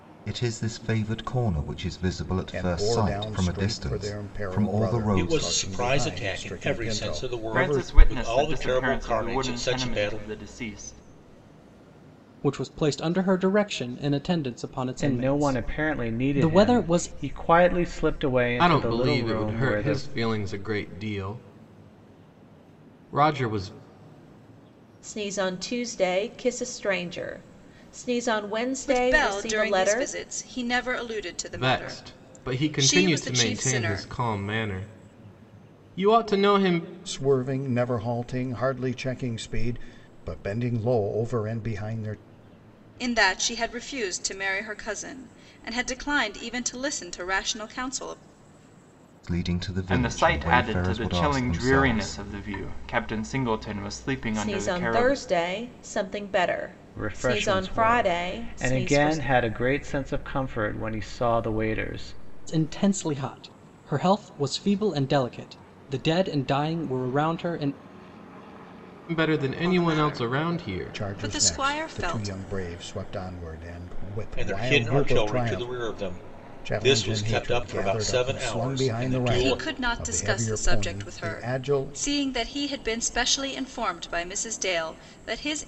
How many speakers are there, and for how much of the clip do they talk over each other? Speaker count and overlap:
9, about 35%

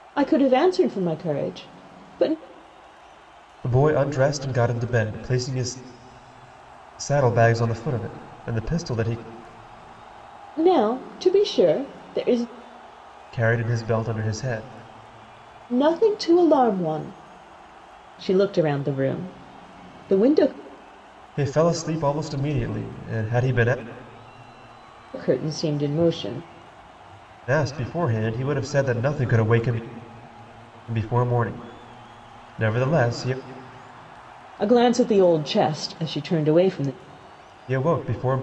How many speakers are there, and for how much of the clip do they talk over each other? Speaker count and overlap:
2, no overlap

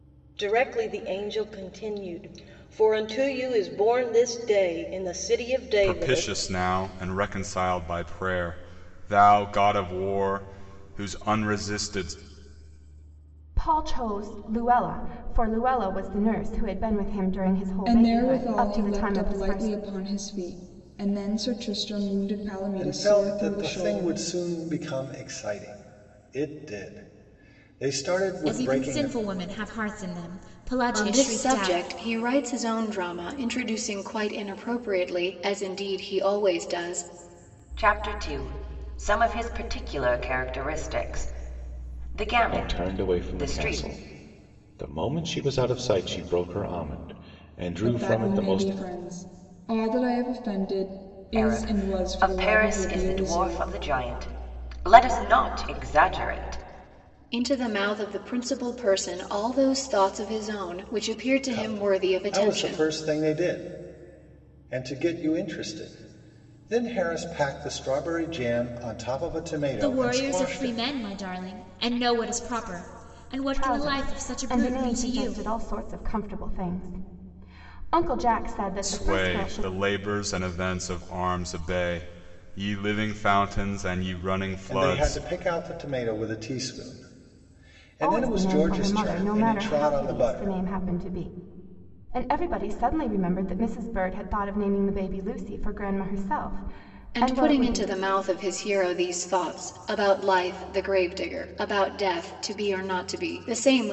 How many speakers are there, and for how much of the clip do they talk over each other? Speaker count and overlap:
9, about 19%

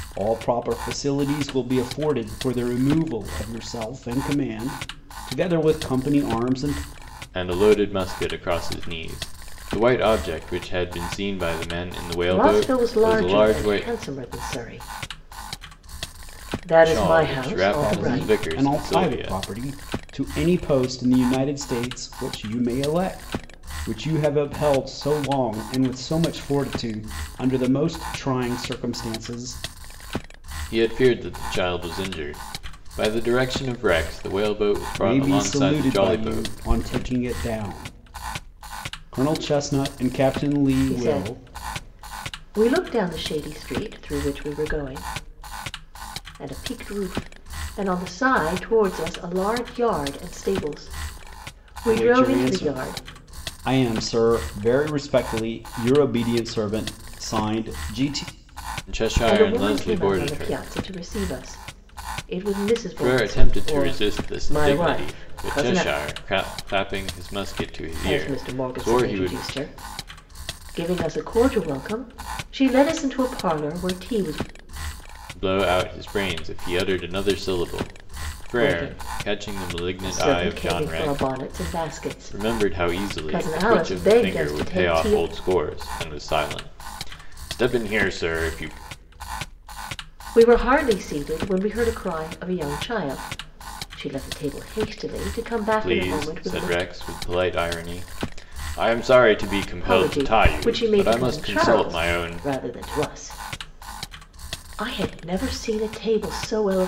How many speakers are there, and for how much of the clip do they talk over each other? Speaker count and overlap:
3, about 22%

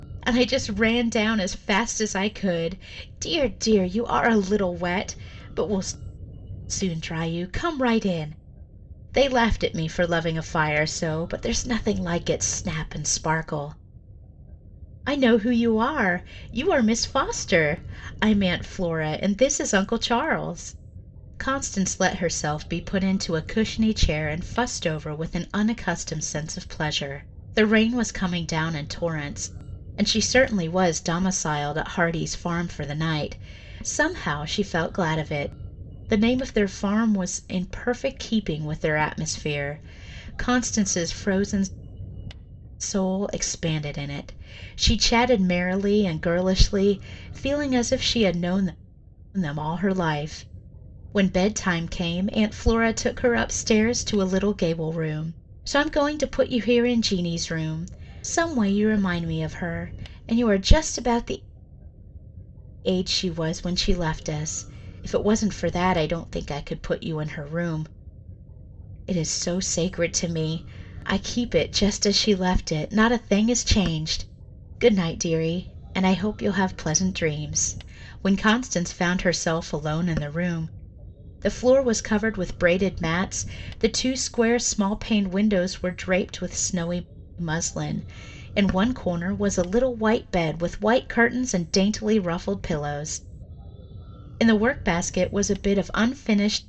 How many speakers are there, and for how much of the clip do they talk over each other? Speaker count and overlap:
1, no overlap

